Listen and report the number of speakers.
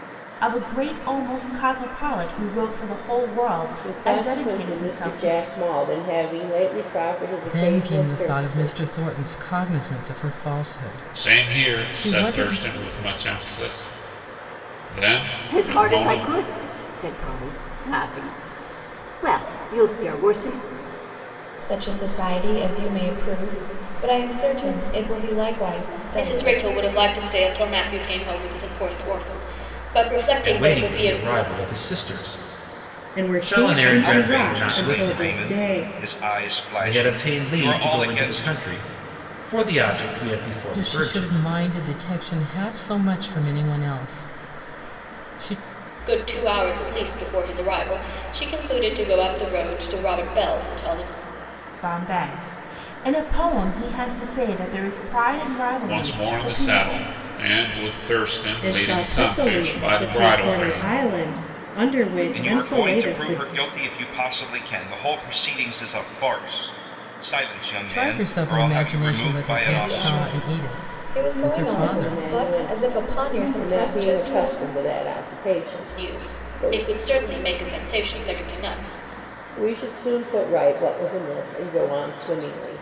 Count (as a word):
ten